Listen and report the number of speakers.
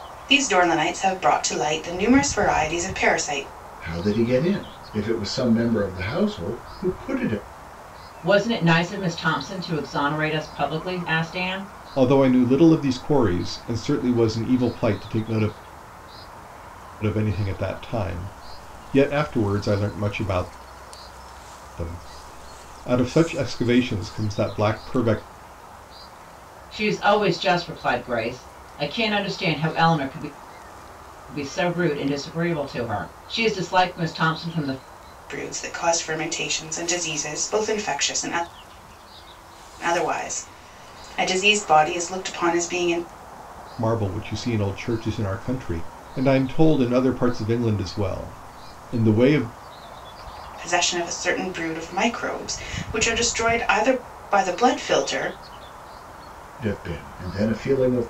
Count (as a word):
four